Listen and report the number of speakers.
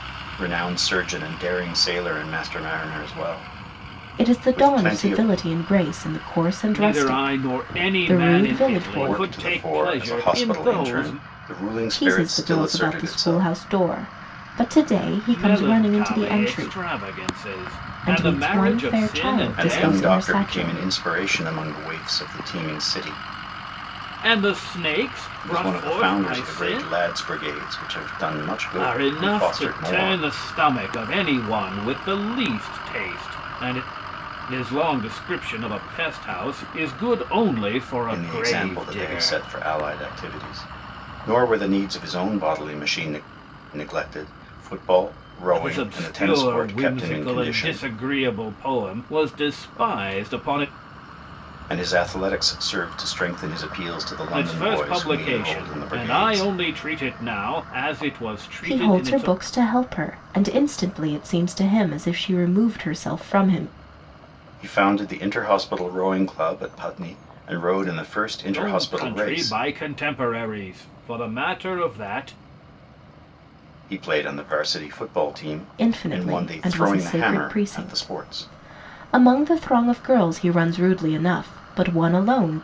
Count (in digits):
3